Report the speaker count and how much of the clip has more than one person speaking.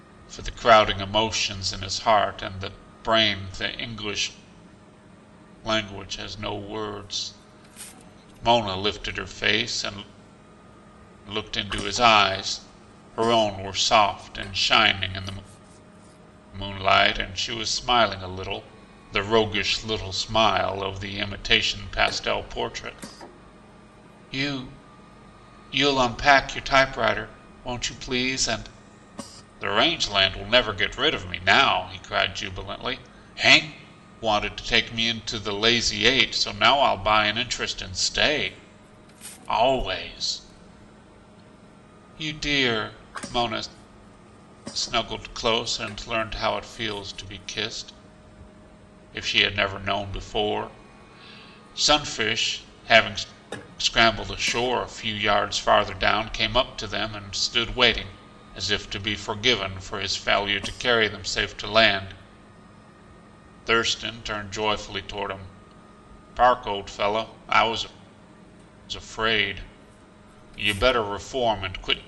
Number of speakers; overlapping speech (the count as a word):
one, no overlap